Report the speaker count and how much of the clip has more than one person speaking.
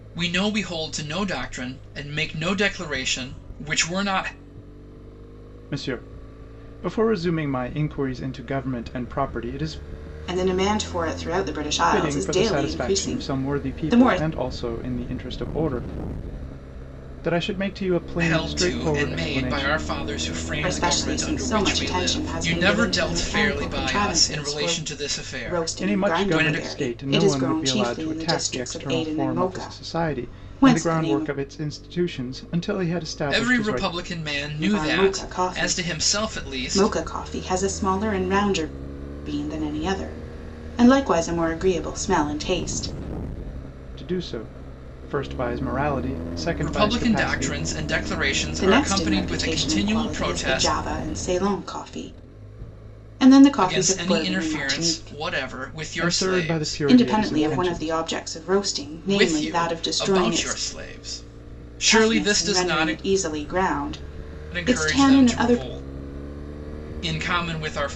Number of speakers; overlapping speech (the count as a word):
three, about 41%